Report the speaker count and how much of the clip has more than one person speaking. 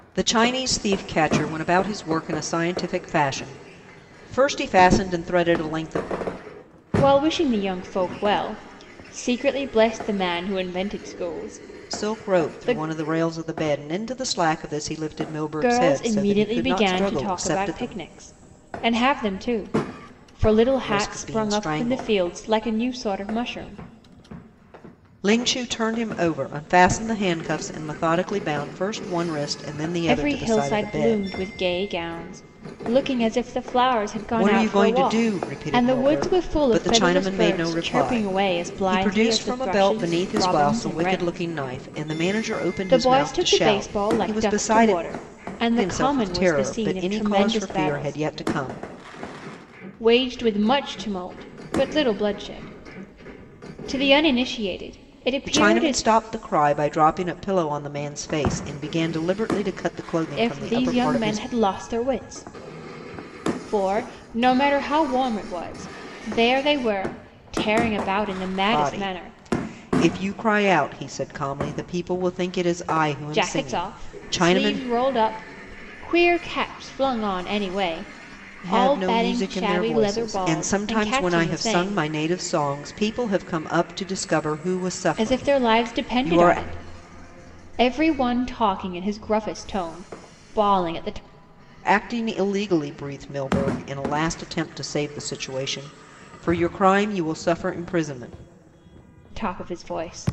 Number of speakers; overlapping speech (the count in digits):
2, about 26%